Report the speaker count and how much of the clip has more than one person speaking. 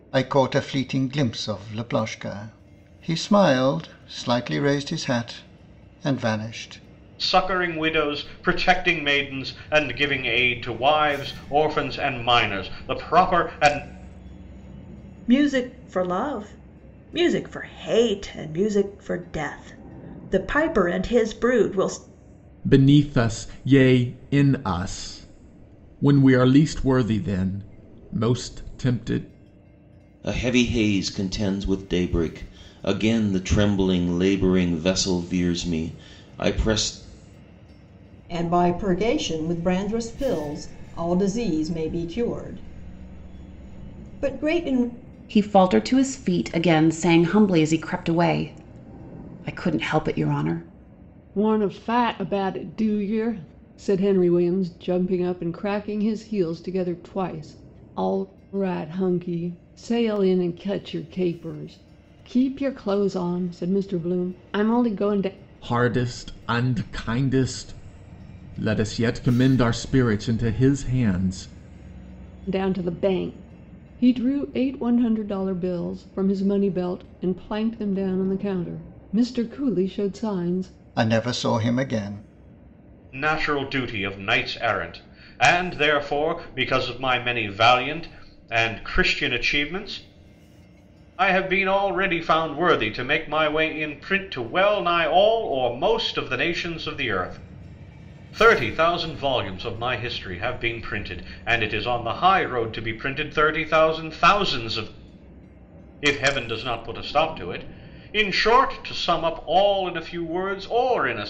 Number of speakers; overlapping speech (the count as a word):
eight, no overlap